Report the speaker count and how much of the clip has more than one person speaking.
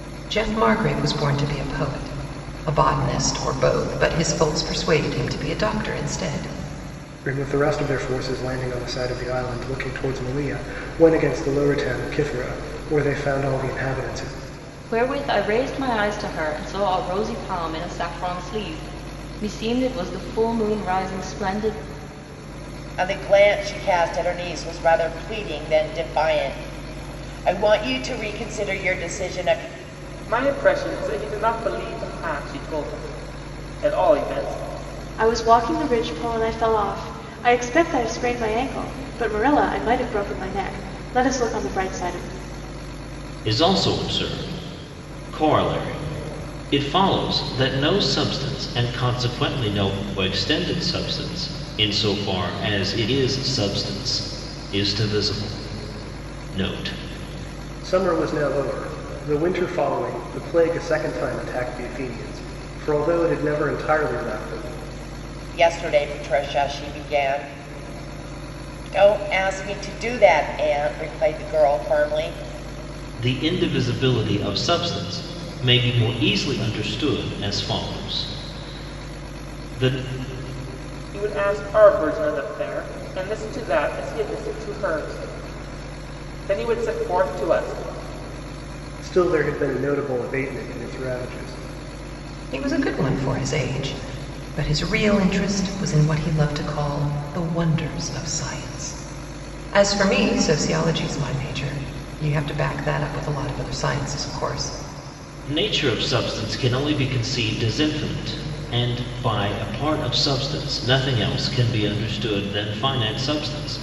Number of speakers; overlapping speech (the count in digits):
7, no overlap